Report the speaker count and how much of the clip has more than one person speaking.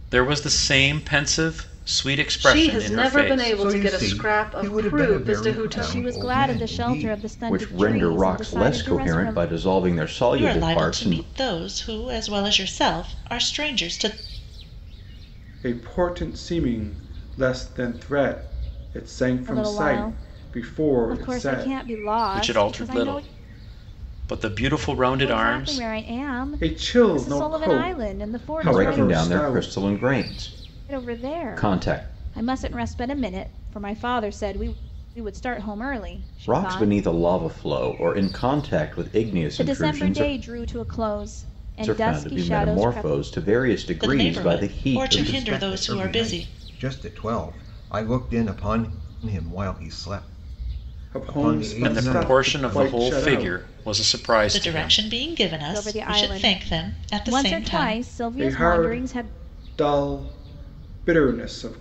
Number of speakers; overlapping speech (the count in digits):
7, about 45%